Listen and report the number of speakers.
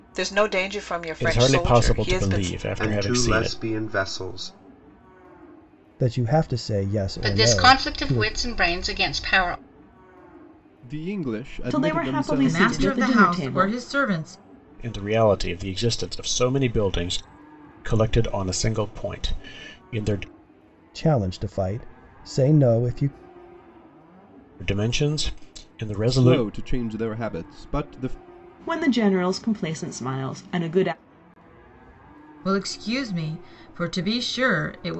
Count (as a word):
eight